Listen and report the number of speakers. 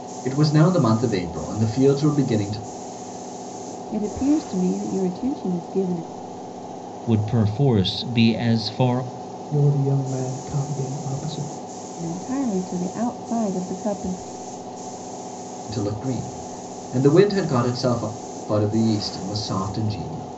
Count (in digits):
4